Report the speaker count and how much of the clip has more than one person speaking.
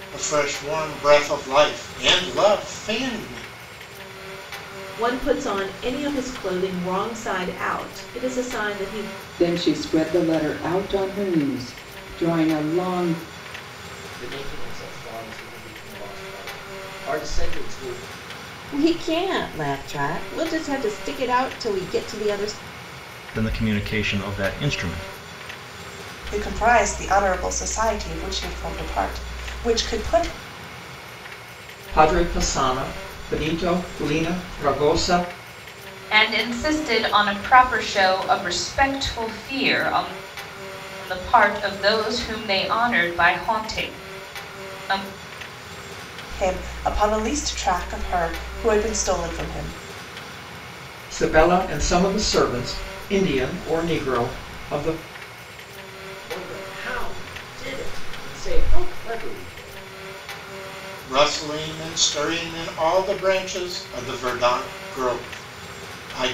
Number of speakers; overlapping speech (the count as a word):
nine, no overlap